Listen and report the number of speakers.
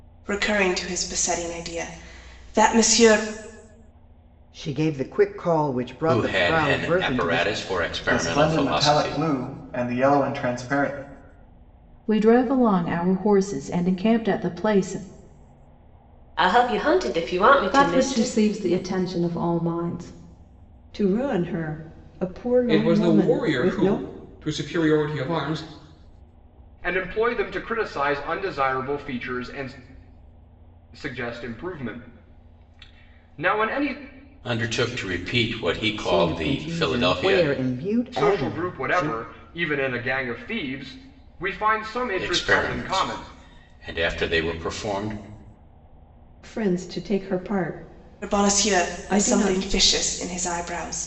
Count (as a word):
ten